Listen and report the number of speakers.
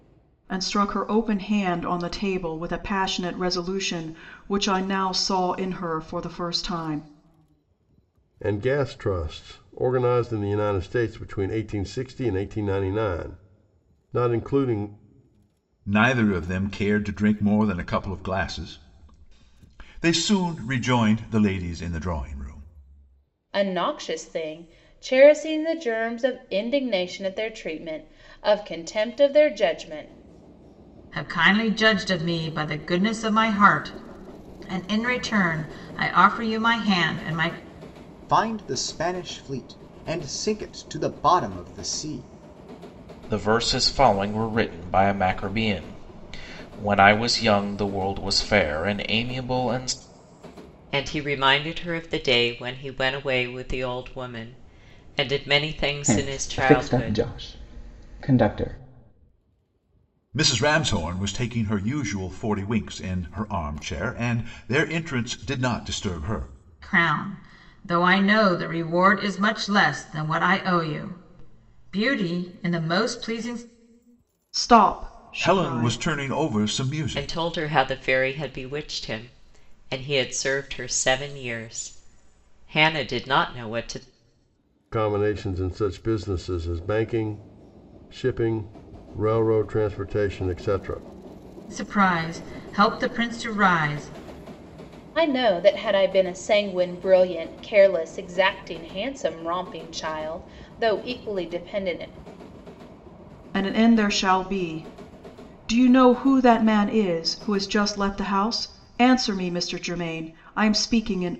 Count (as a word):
nine